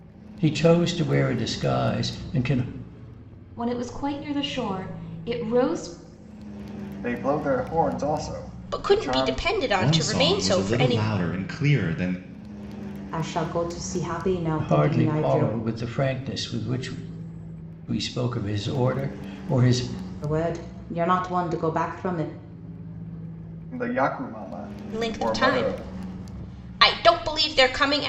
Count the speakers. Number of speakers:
six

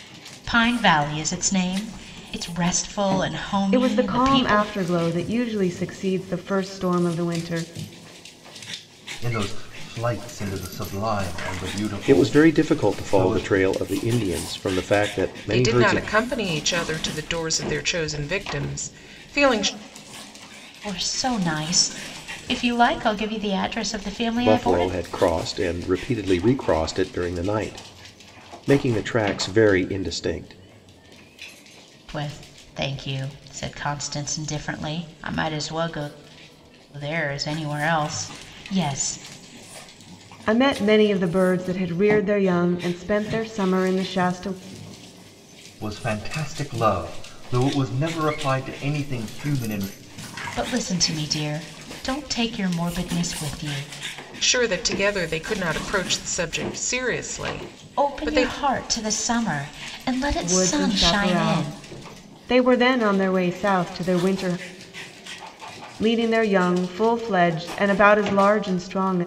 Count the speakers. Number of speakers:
five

